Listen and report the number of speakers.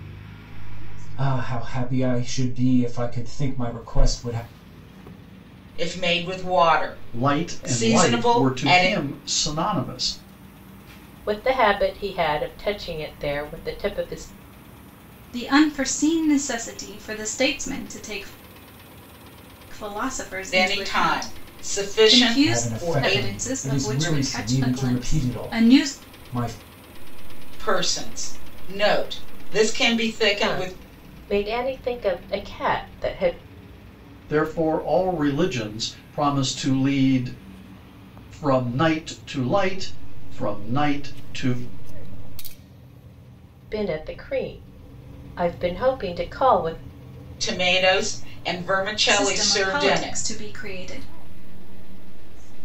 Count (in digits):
6